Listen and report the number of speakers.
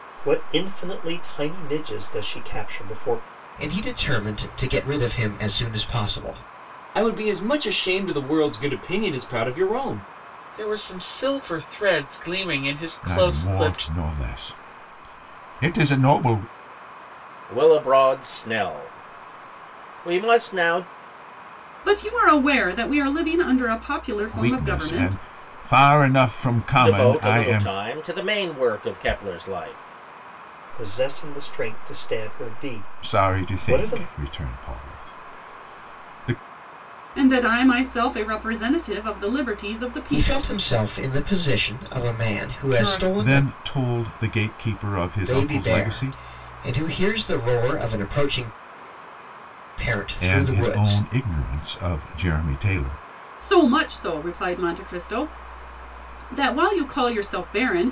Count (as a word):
seven